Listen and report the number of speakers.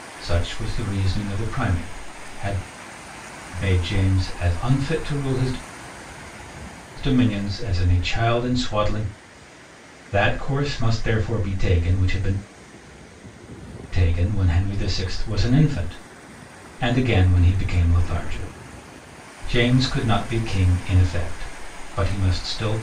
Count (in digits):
1